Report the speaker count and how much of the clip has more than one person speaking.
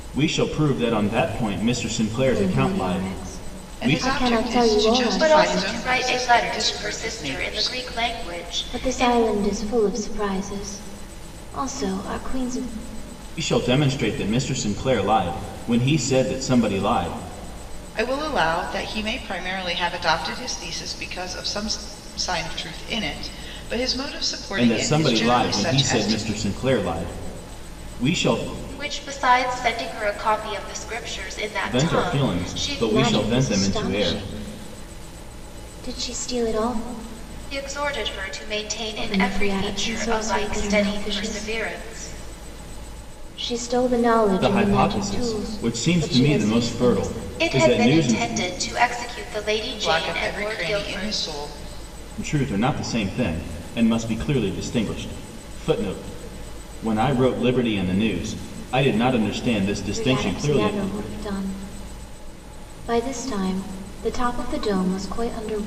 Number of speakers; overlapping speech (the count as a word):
four, about 29%